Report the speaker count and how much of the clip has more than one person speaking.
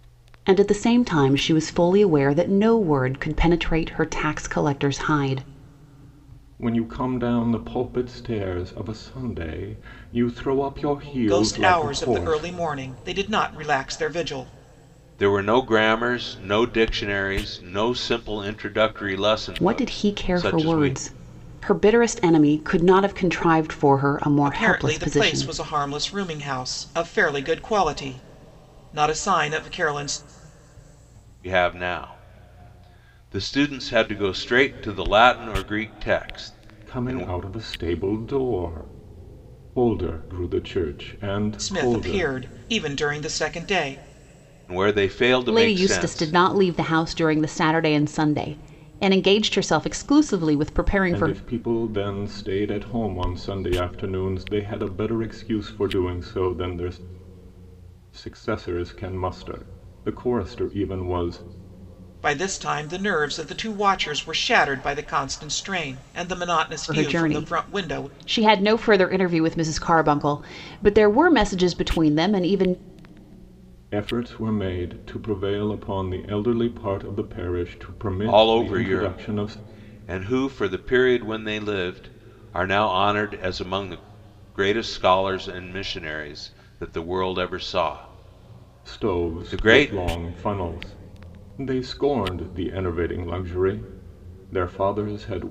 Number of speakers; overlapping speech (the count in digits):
4, about 10%